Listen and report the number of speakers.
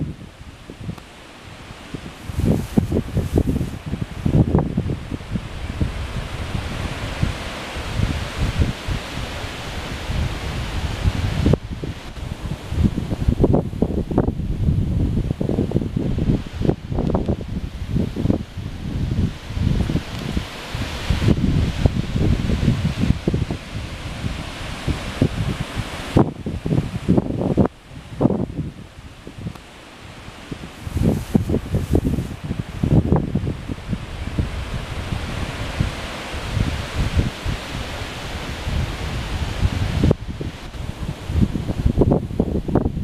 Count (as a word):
zero